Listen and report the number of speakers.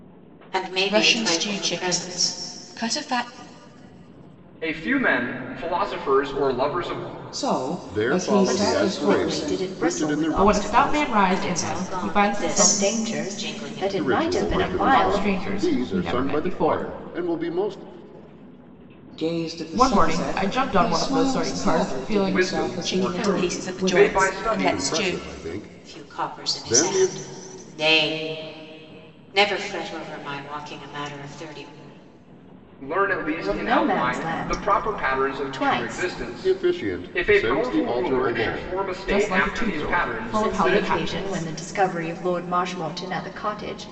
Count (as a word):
seven